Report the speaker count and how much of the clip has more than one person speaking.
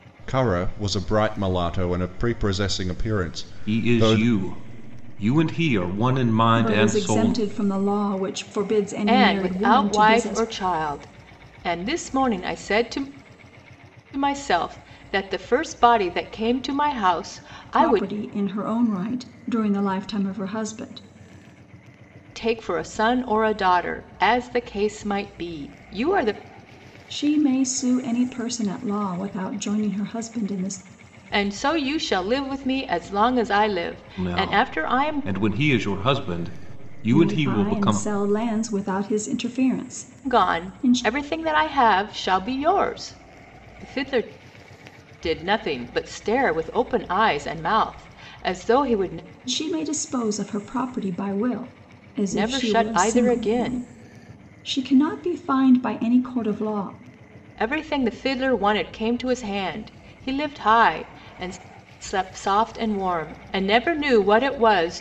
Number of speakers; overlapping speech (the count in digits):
4, about 12%